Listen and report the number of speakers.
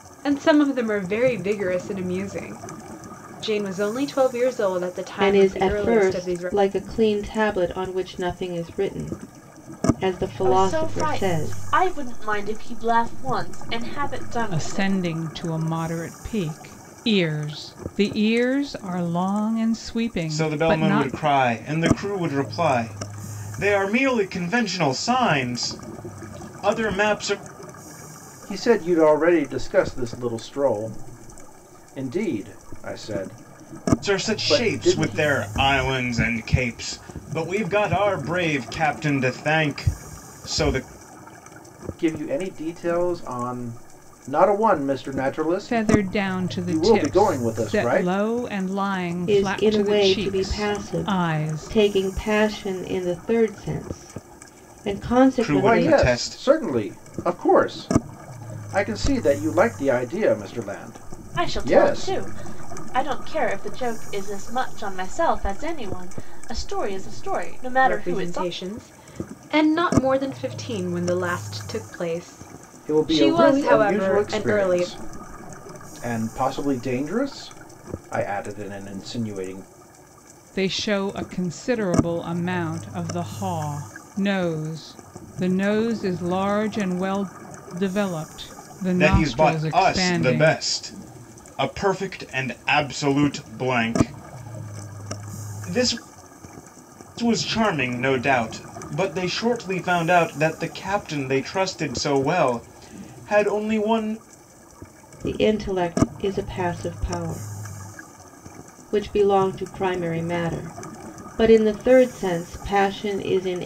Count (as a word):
six